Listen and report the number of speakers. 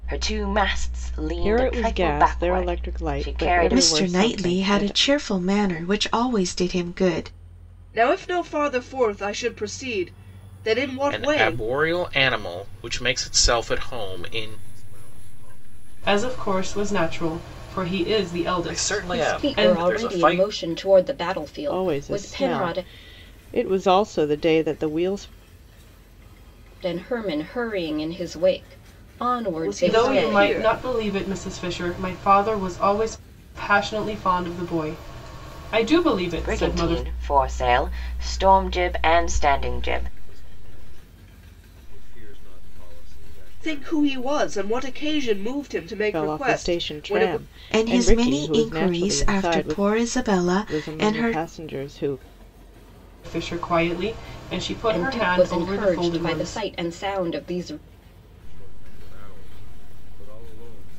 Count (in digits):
9